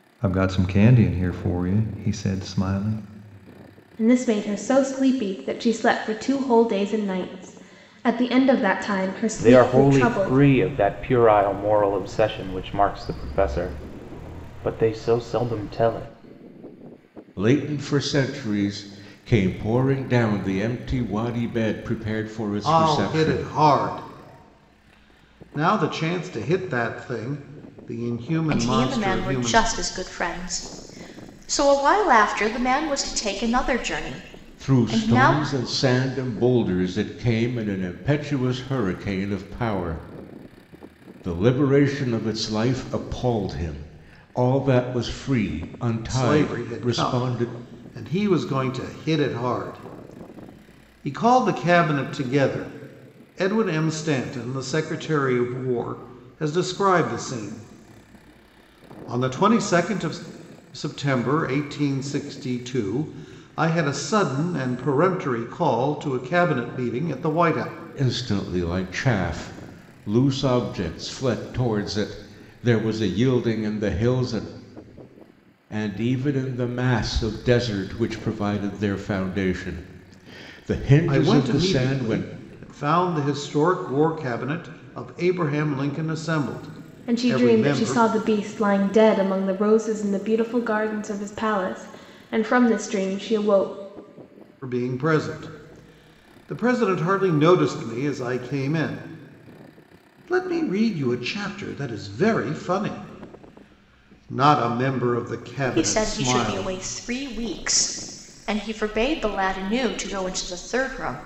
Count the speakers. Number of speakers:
6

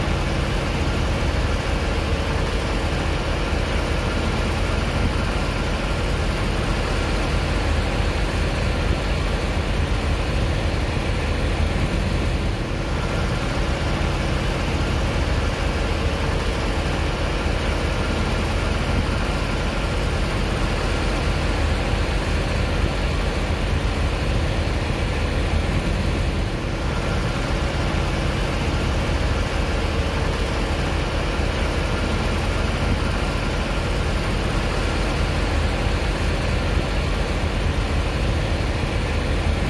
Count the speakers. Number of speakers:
0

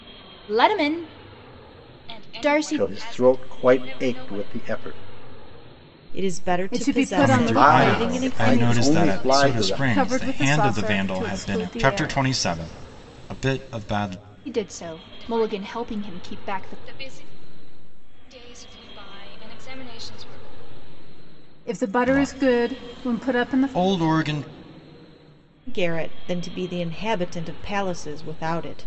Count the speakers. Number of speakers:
6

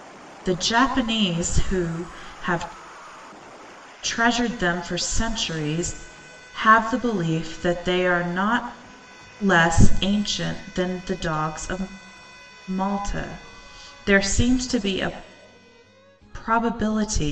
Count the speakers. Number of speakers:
1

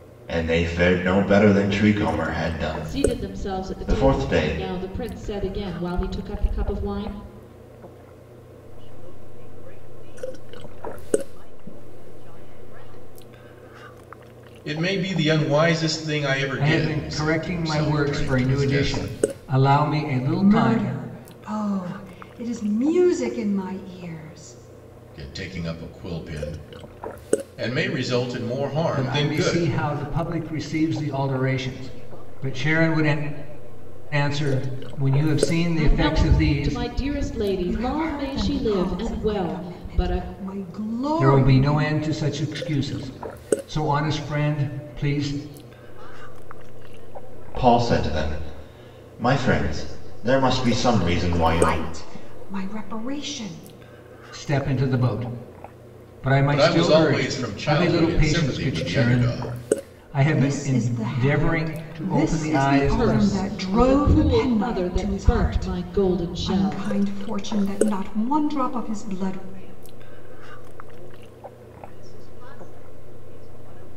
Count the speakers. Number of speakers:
6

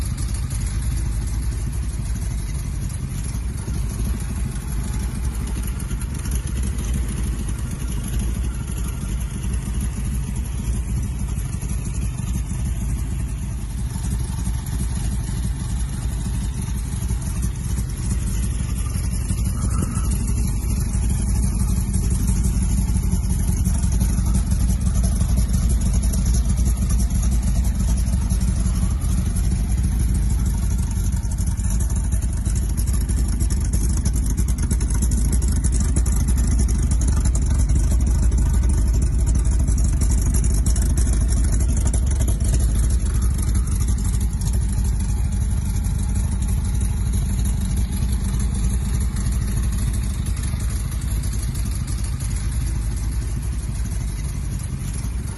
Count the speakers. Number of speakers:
0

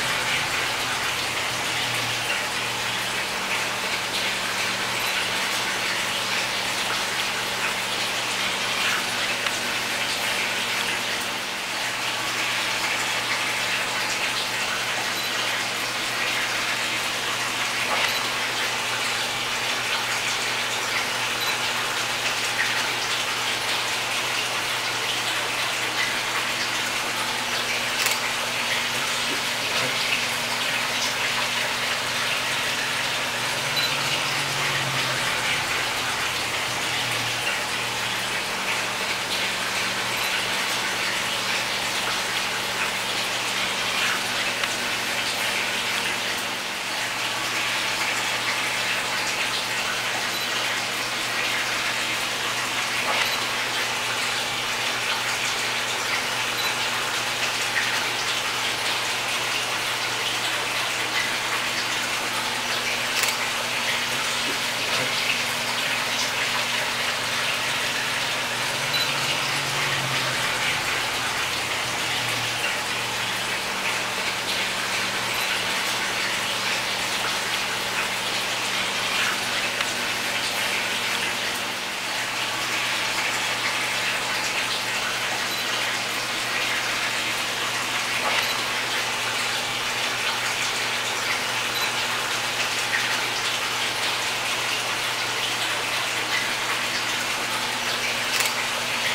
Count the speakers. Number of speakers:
0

